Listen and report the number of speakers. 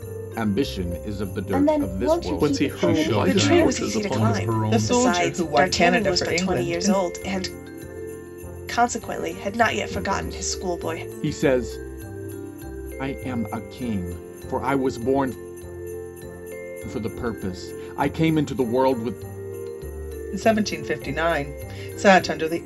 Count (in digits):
6